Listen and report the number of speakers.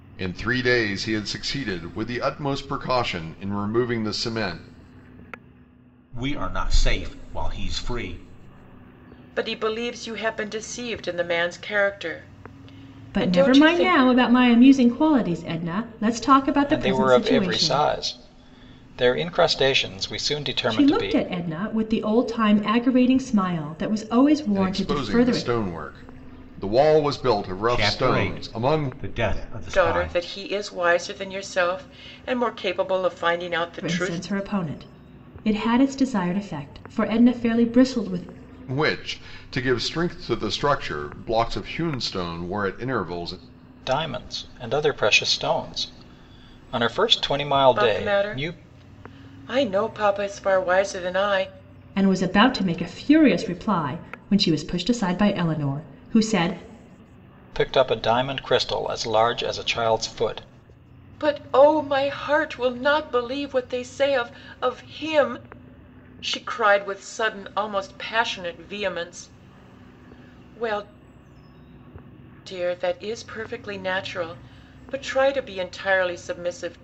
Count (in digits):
5